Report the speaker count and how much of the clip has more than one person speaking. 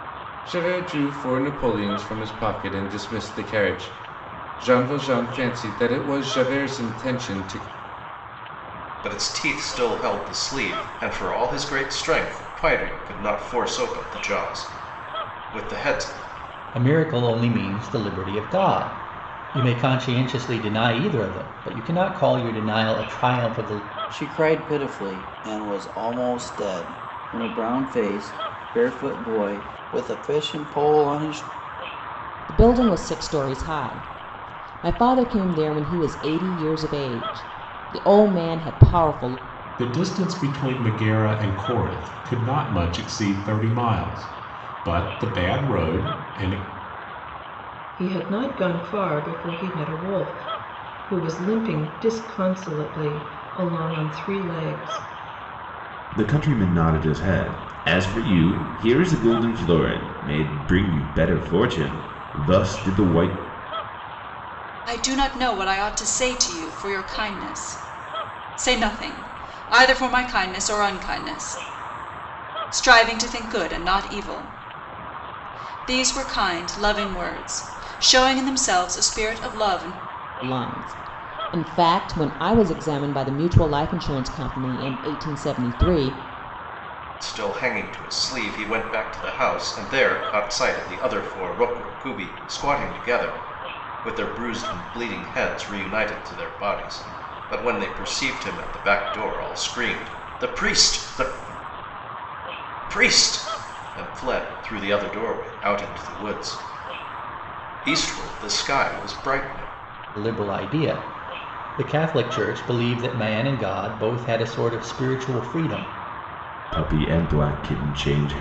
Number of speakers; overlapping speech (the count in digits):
9, no overlap